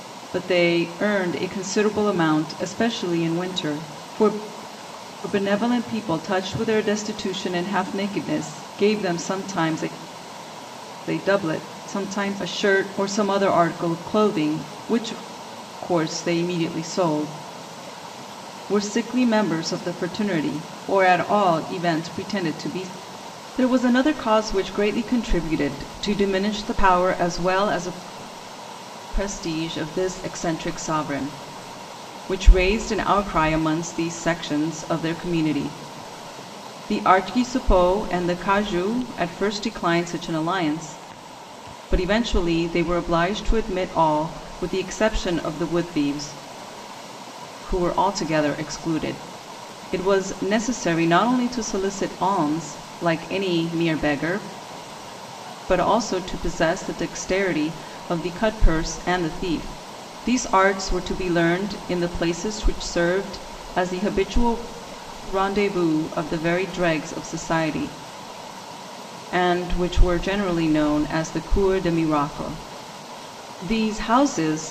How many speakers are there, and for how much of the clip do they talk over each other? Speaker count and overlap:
one, no overlap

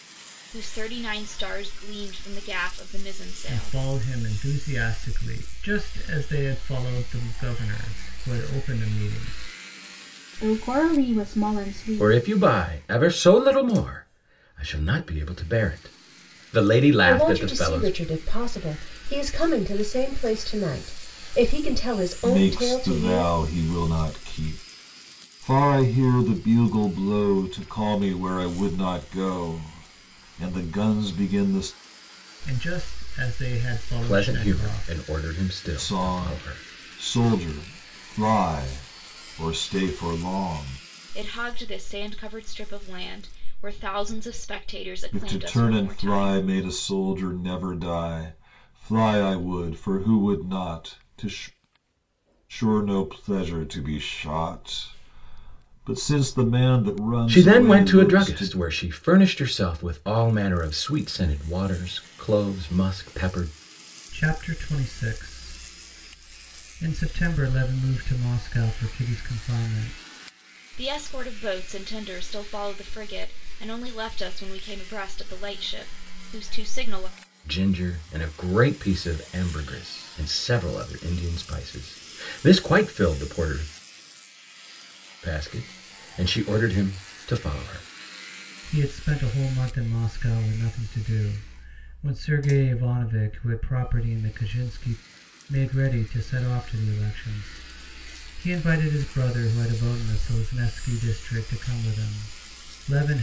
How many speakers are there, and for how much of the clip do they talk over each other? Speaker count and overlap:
six, about 7%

